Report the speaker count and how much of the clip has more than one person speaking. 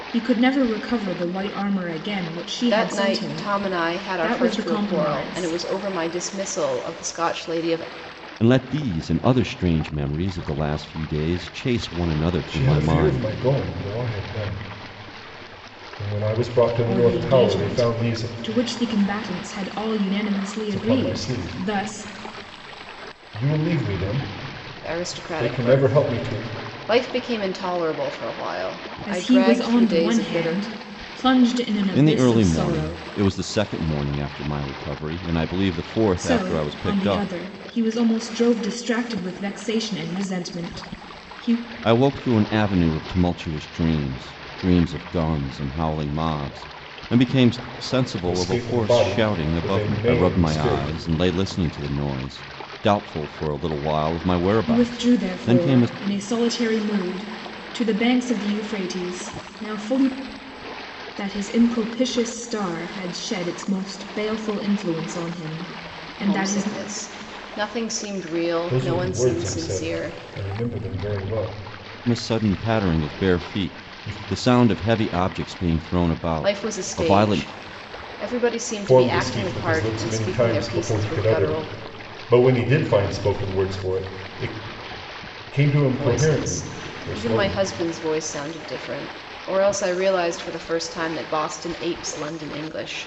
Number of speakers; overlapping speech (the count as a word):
four, about 28%